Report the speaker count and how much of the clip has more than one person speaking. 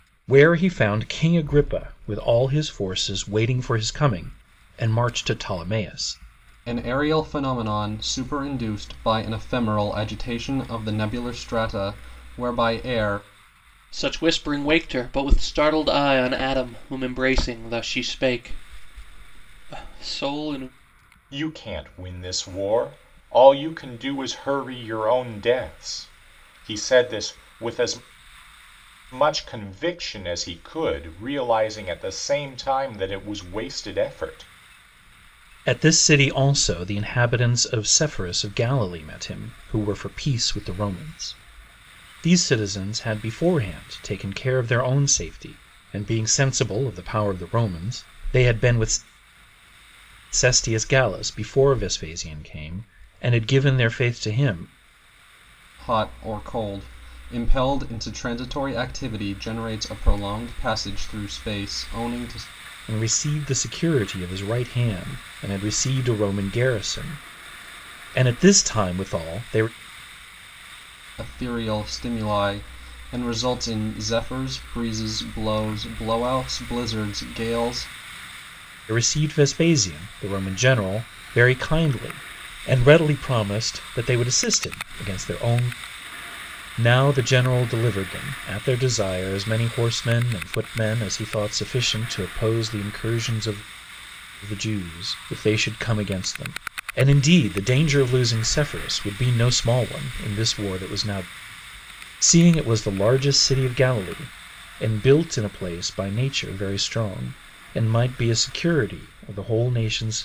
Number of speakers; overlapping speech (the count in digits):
4, no overlap